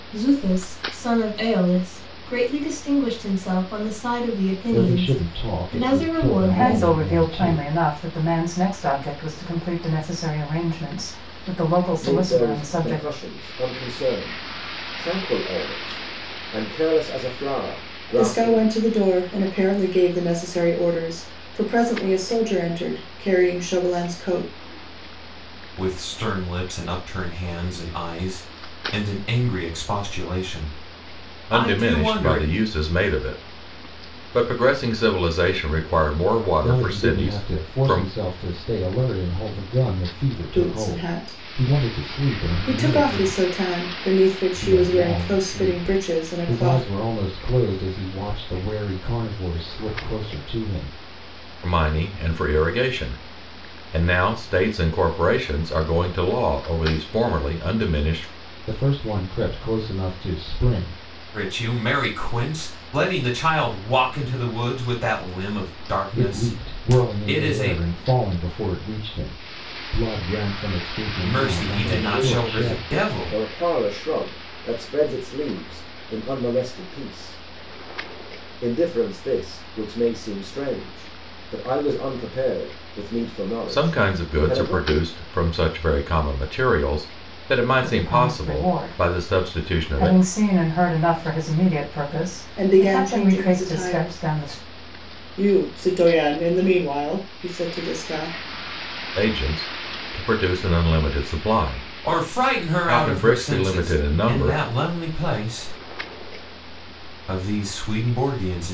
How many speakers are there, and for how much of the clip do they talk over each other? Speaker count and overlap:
7, about 23%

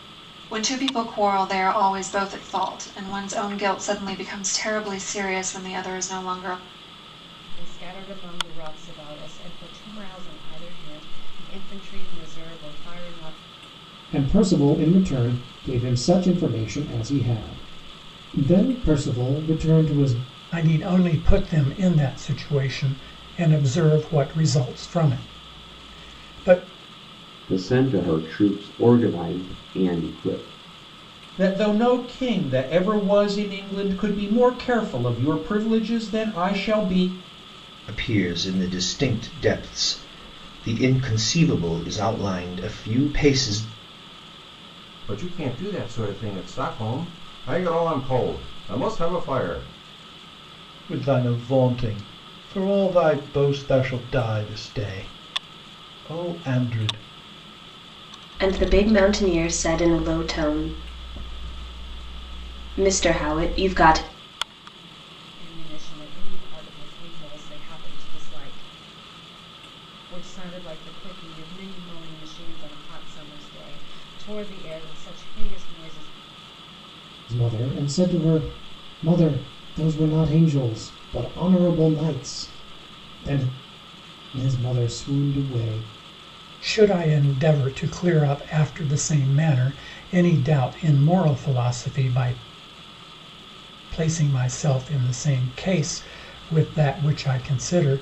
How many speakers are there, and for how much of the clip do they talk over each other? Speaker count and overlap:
10, no overlap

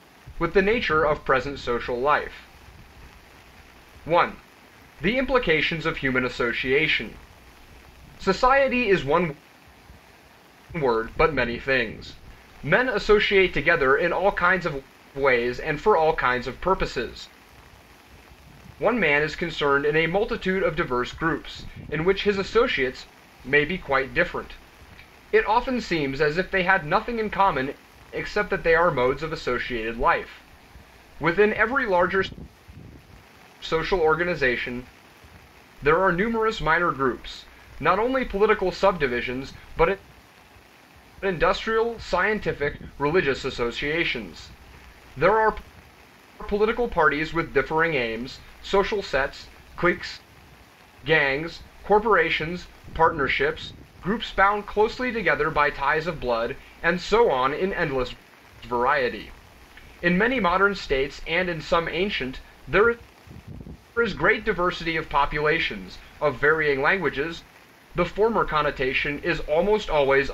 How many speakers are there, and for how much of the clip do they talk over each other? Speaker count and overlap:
1, no overlap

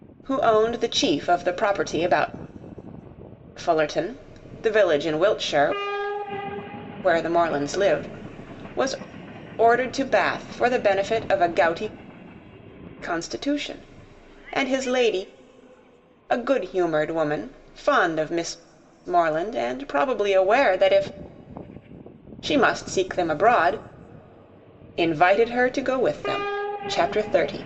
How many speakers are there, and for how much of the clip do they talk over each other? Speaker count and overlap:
1, no overlap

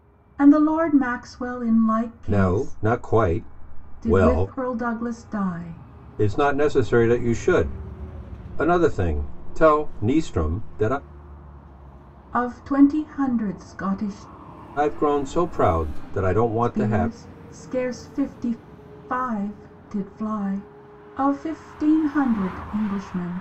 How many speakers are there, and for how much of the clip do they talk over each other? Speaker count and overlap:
2, about 7%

